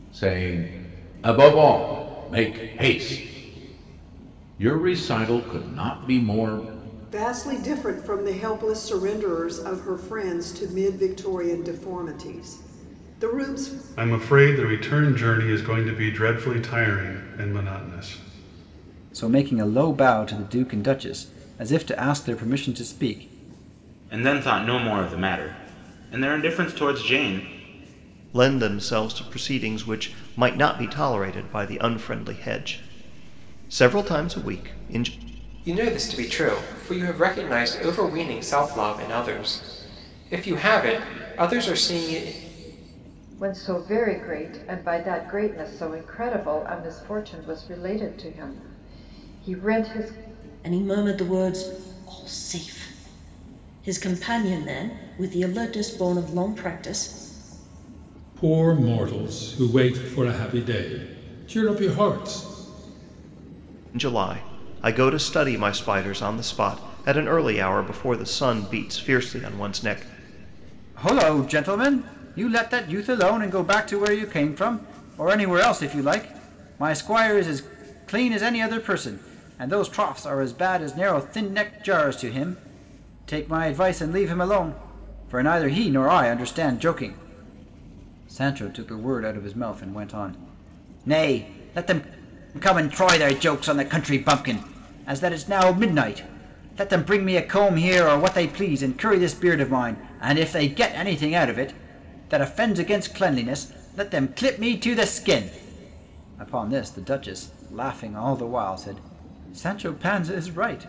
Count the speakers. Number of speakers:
10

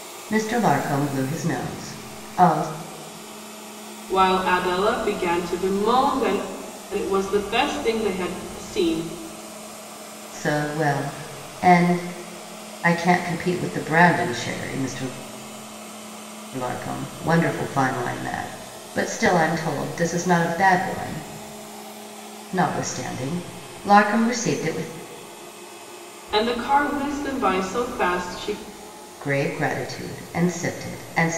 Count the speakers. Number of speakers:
2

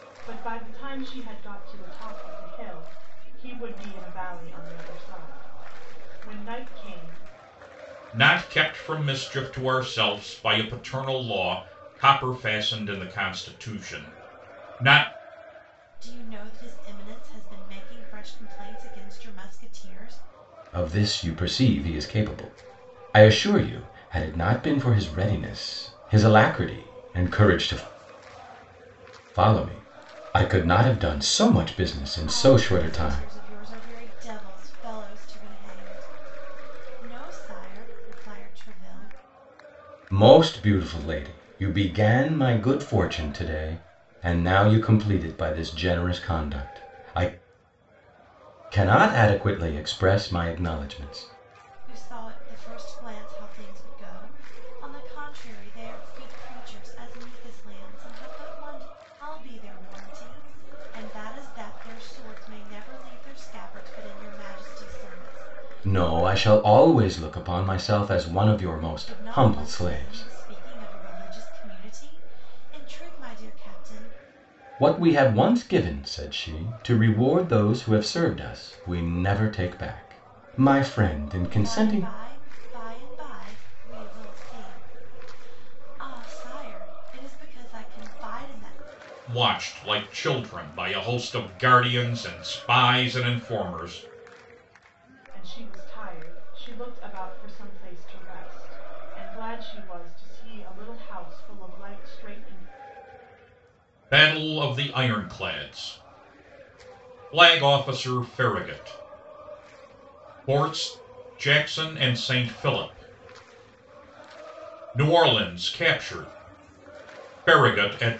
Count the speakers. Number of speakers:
4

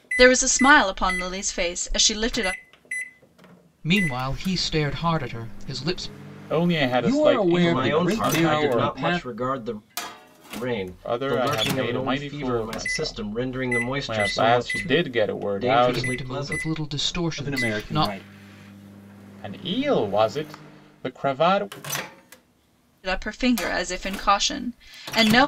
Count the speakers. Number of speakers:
5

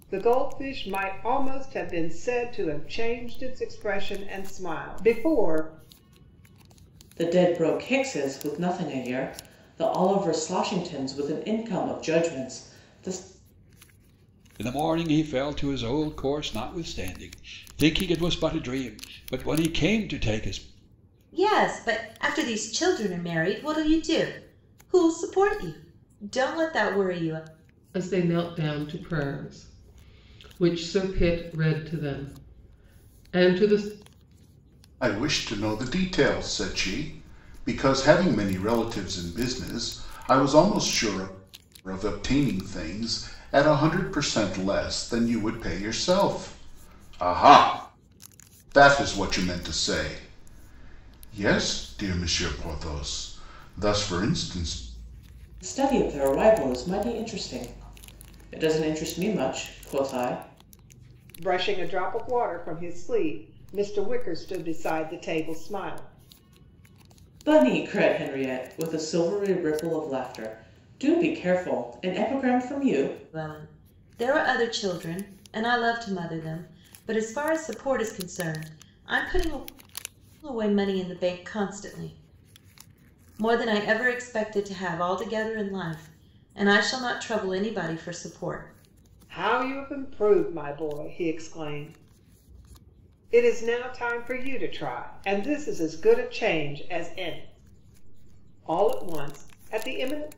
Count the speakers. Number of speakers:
6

